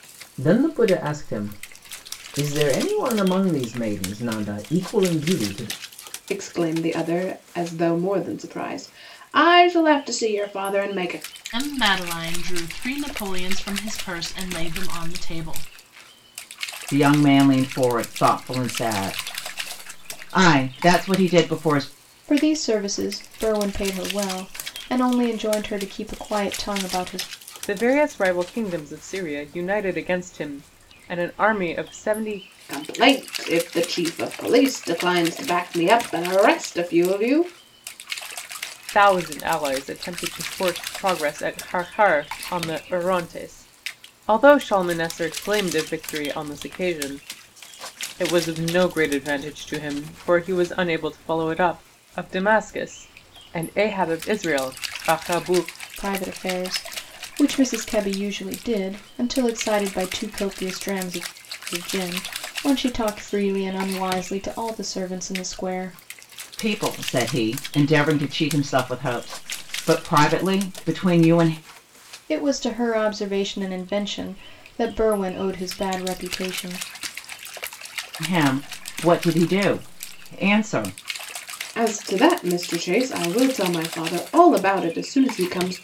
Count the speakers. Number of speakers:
six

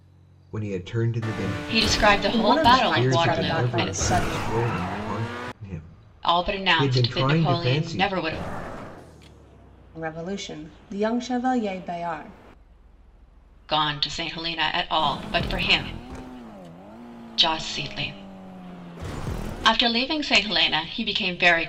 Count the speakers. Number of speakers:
three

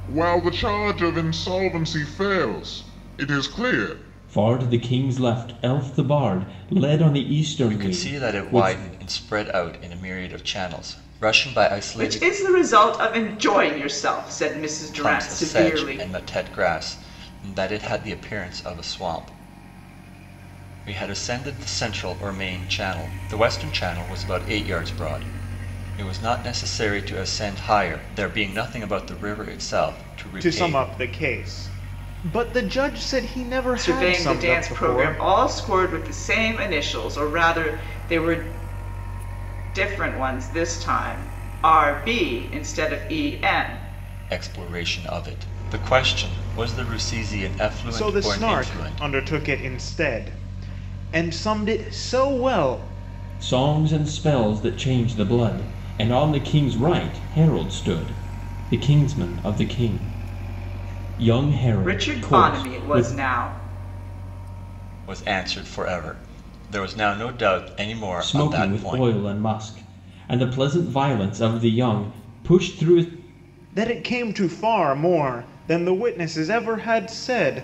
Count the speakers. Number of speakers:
four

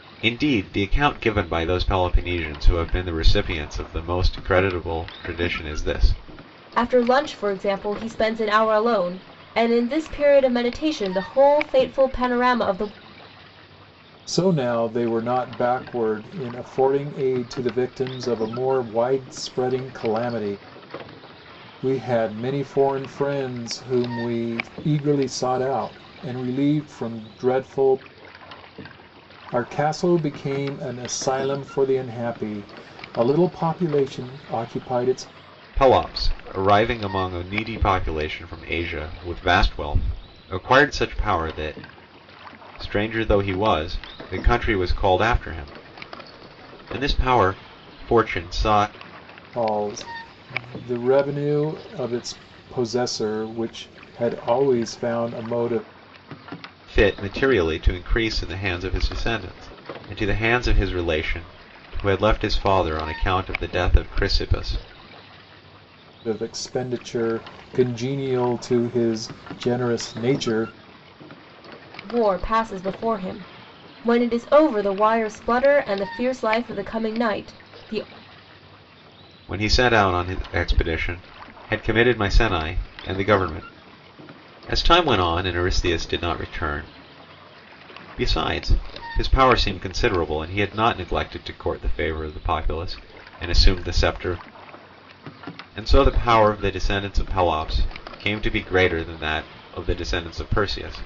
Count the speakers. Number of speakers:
three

